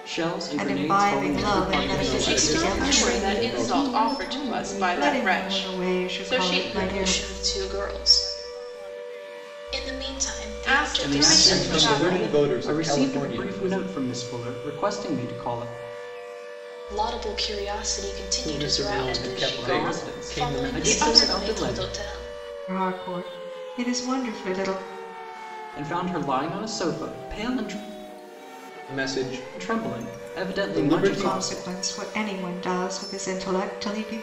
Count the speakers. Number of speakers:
six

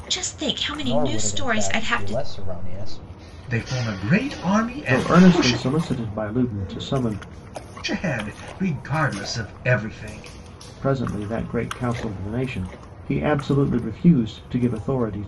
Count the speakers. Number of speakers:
four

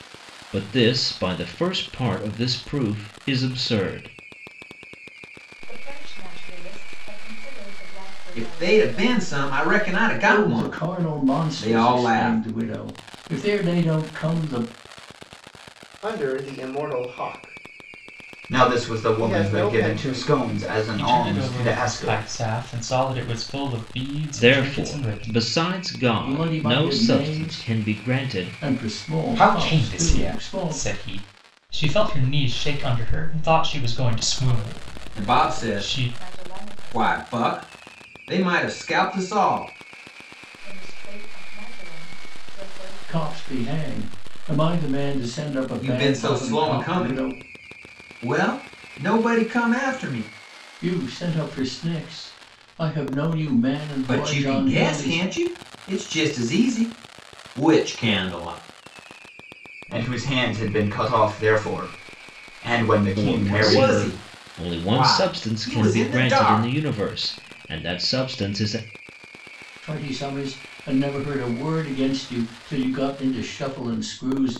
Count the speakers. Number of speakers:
seven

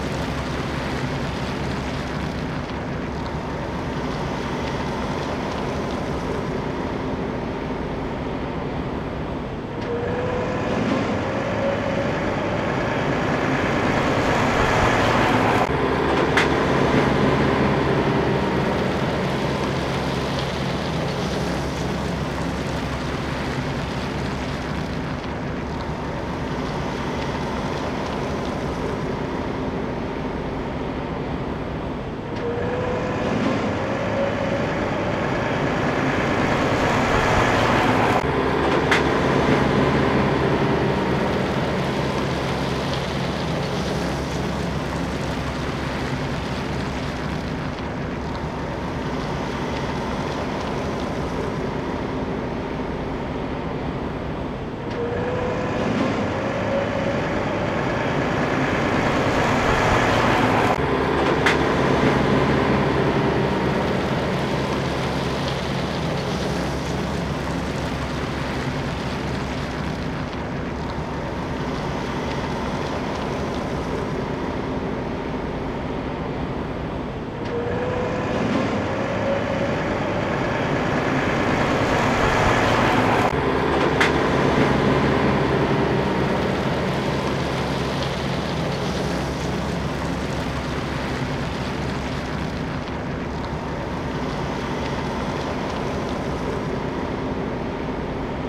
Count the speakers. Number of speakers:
zero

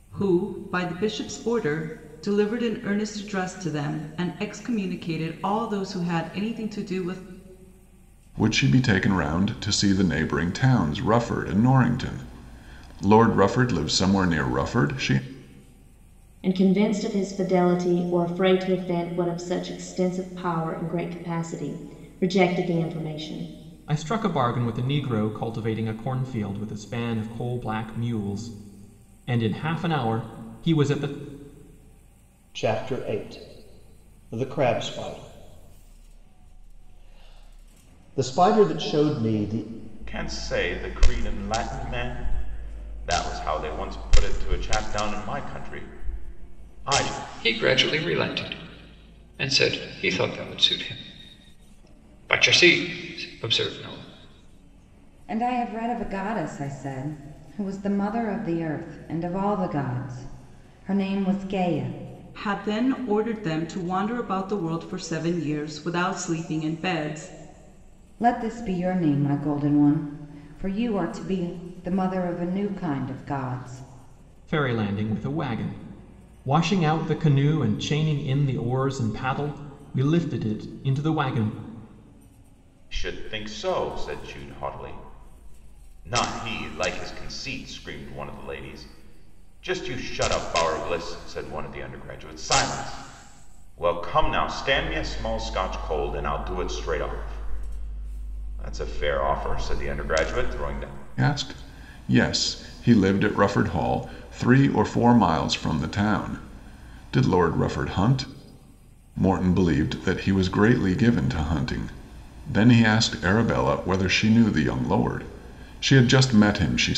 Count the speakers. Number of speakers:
eight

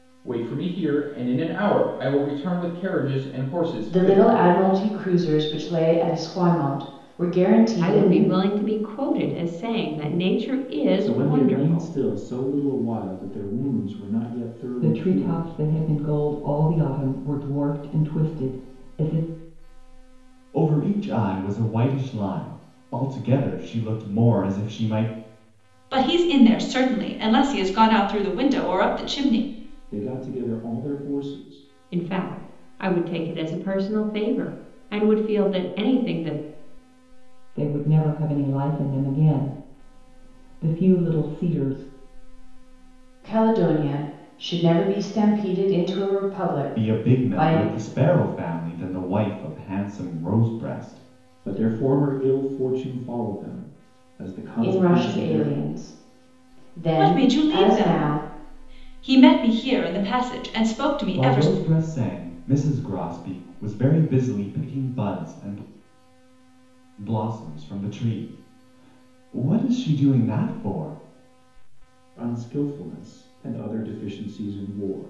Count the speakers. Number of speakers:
seven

